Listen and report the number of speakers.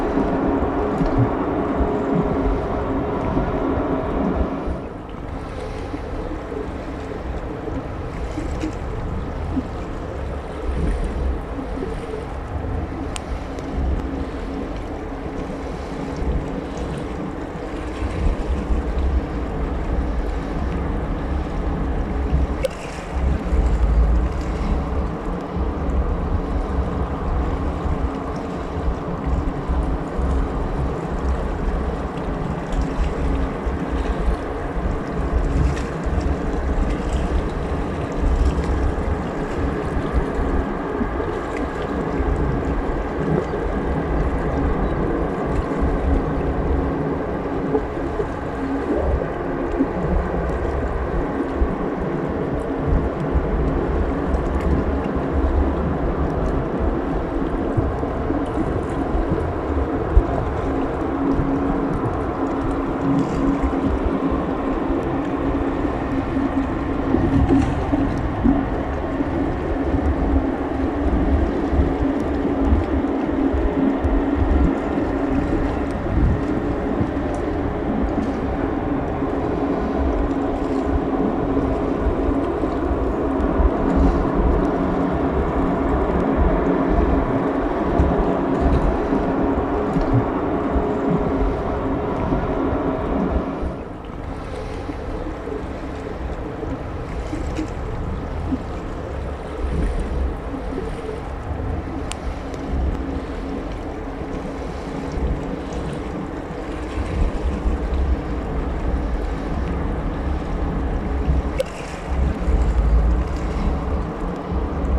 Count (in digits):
0